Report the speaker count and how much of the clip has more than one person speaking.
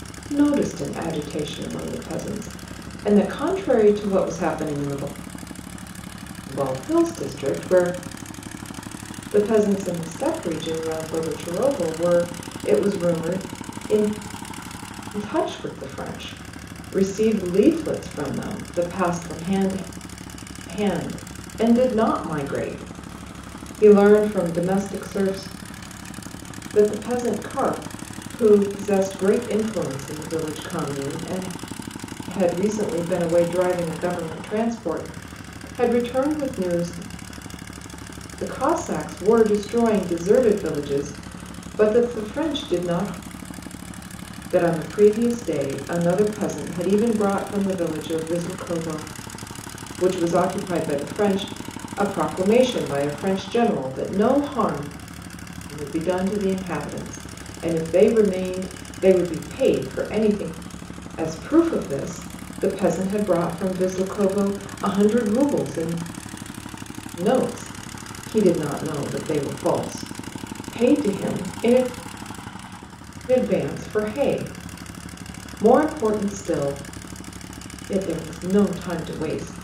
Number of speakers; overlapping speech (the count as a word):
one, no overlap